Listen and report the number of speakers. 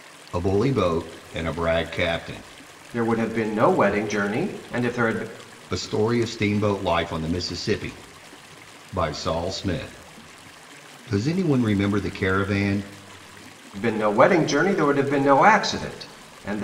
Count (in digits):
2